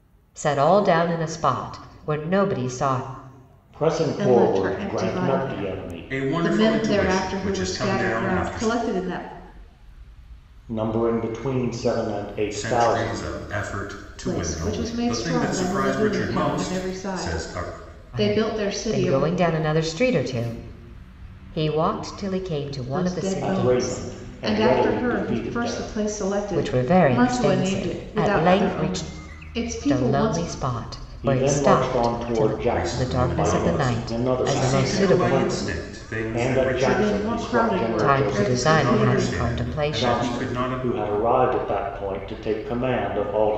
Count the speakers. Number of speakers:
4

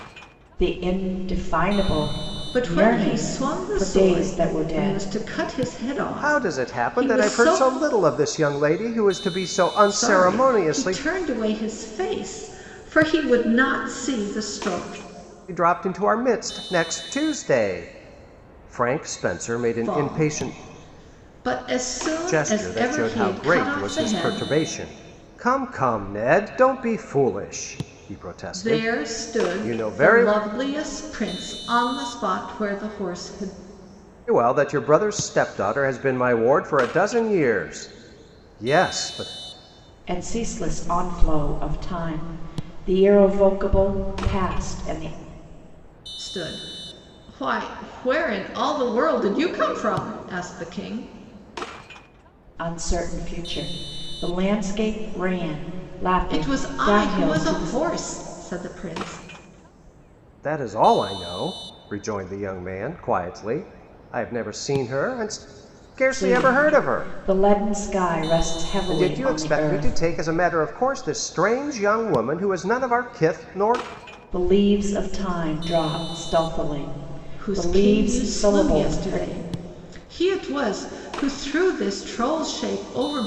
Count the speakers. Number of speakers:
3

